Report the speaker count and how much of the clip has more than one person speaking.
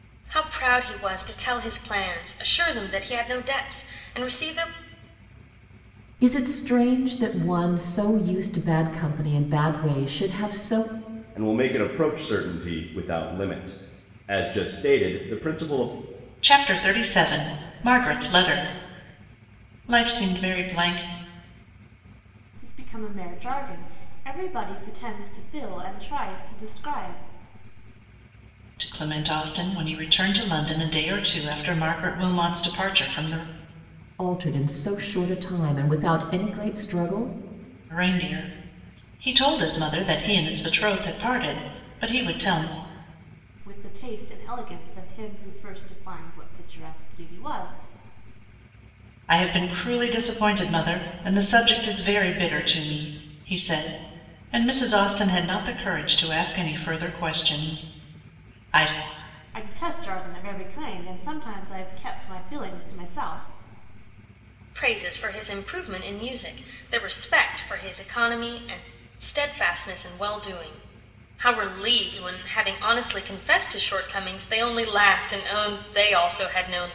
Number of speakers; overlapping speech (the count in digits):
5, no overlap